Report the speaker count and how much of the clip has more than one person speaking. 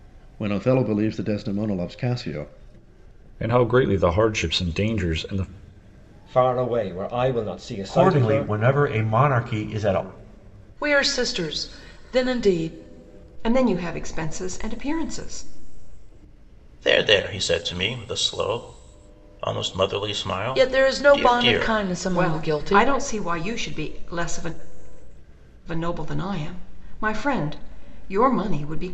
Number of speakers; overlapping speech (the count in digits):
7, about 9%